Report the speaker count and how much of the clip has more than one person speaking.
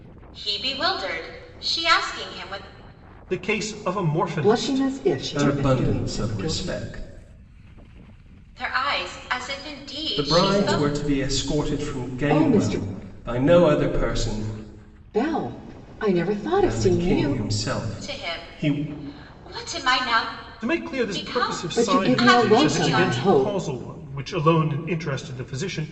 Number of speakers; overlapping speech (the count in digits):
4, about 36%